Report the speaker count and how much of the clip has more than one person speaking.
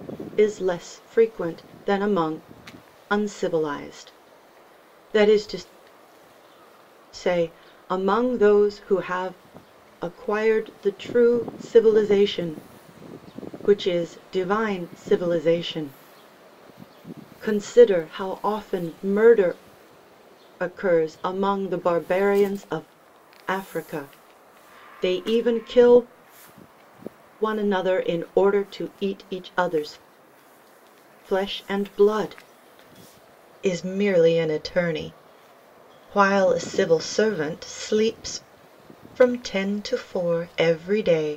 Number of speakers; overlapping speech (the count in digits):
1, no overlap